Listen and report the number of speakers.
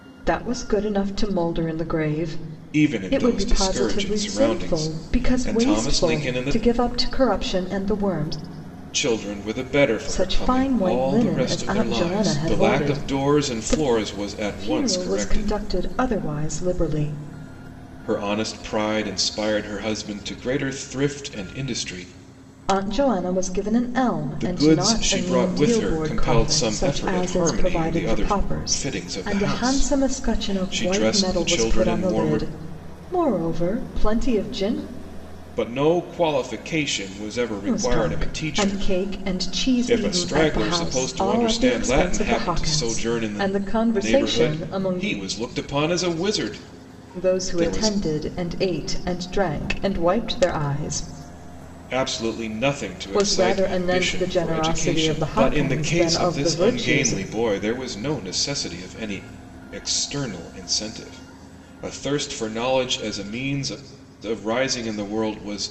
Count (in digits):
2